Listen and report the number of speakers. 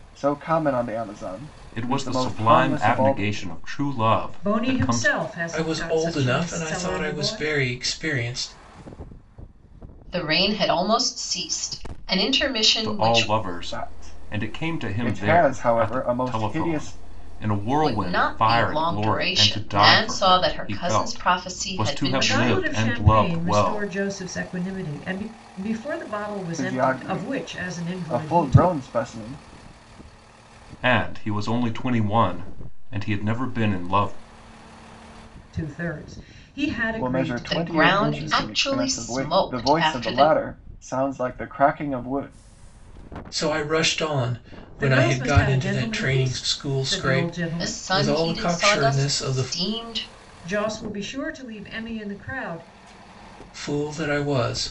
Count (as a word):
five